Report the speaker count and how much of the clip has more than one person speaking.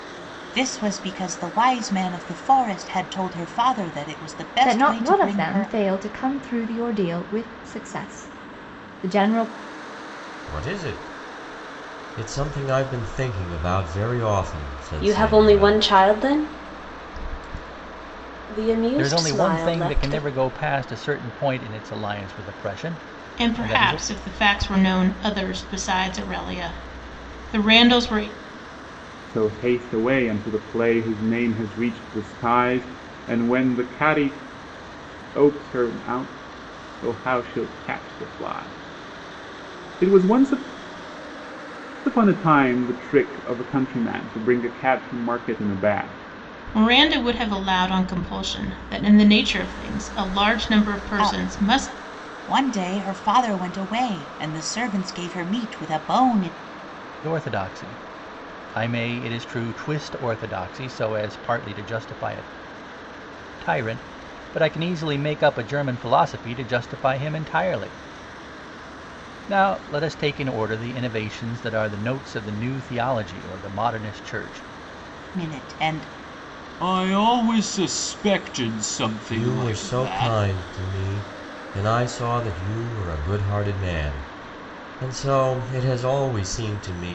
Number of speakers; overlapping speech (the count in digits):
7, about 7%